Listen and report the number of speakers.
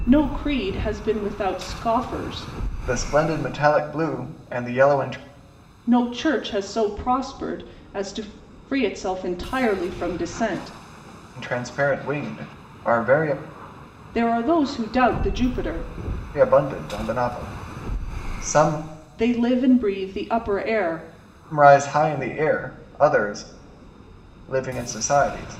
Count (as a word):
two